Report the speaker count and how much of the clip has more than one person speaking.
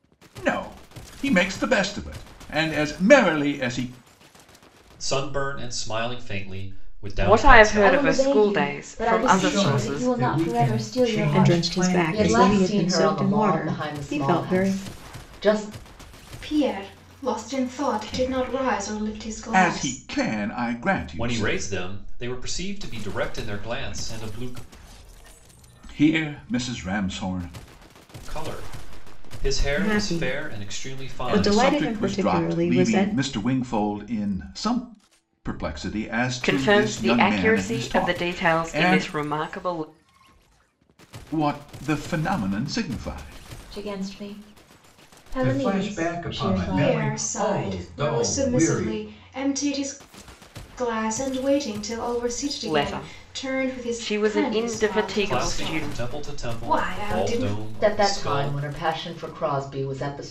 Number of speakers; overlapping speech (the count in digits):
8, about 44%